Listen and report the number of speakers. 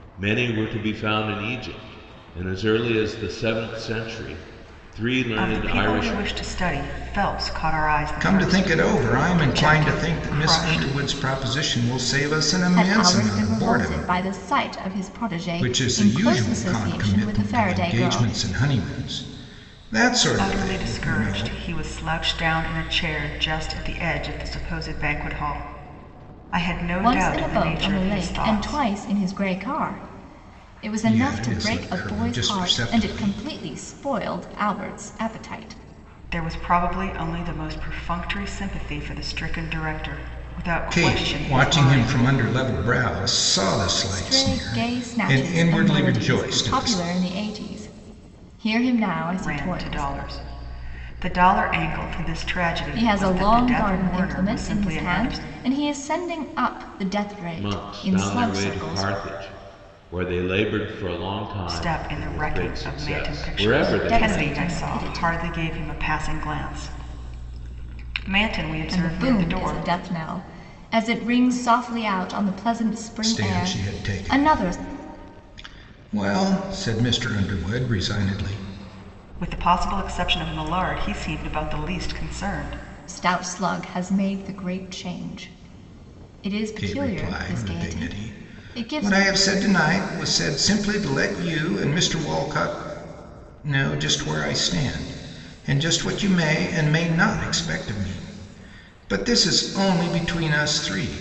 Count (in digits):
4